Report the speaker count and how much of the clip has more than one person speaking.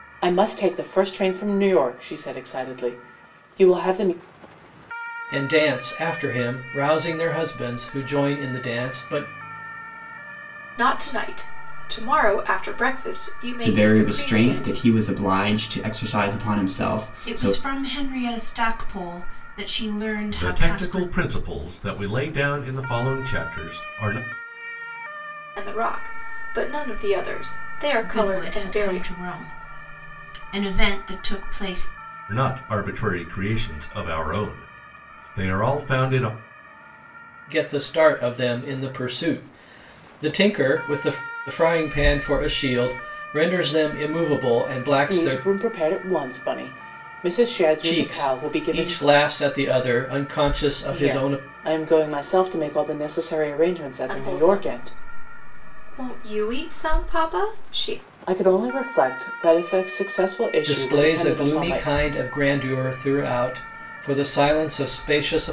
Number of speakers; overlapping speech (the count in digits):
6, about 12%